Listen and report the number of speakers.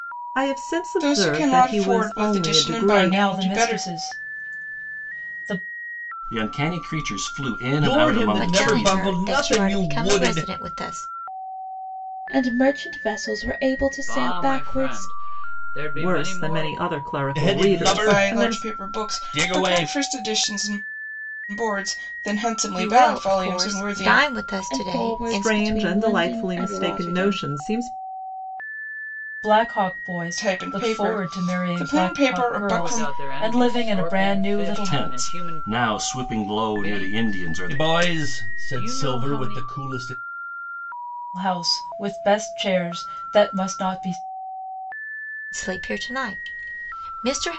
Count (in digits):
8